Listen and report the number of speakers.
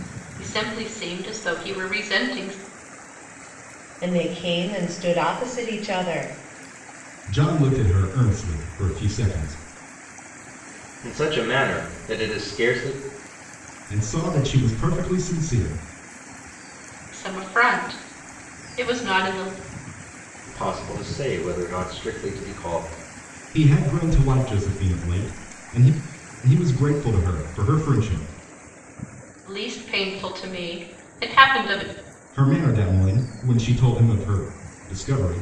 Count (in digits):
4